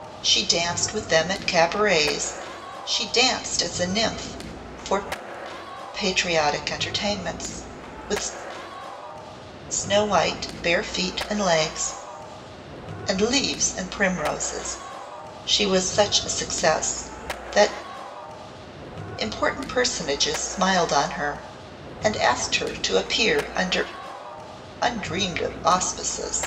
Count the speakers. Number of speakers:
1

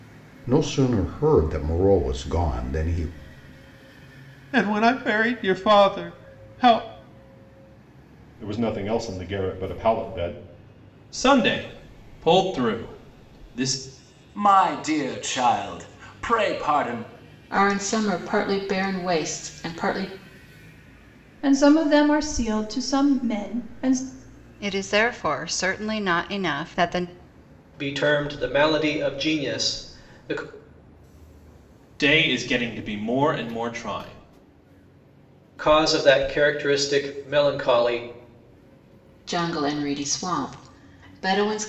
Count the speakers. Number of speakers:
9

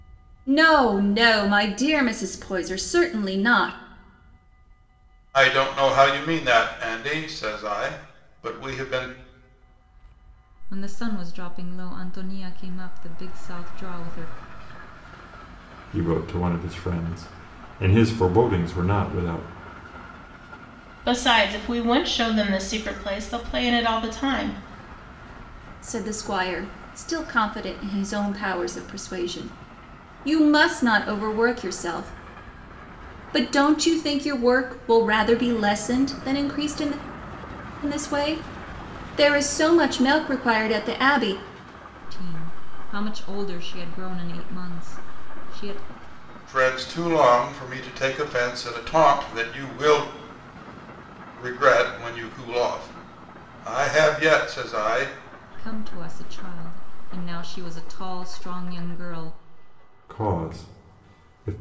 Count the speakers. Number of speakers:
5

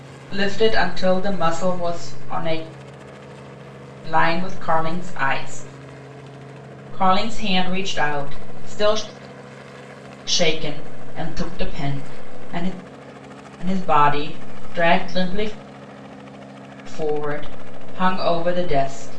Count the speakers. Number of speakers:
1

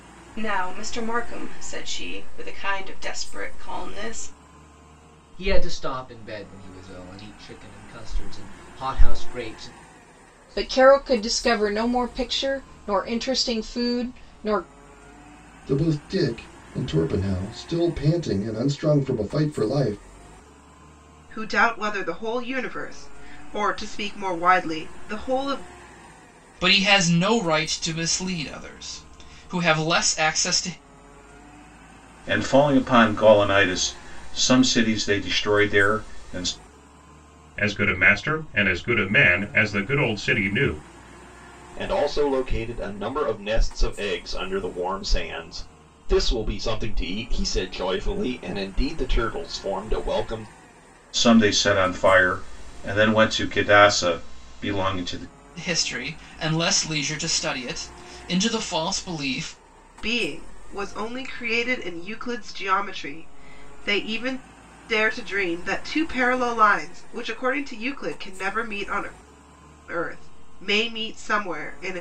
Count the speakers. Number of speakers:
9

